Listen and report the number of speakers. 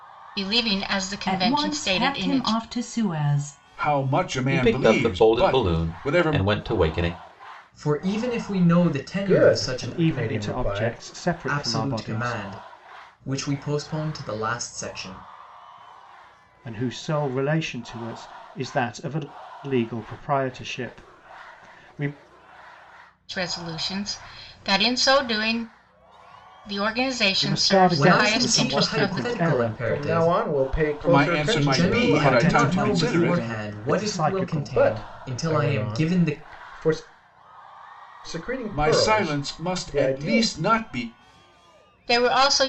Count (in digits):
7